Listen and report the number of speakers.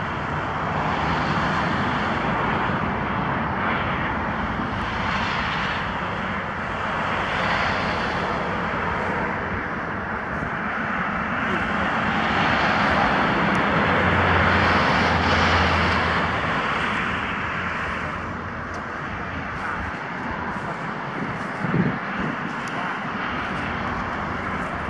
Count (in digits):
0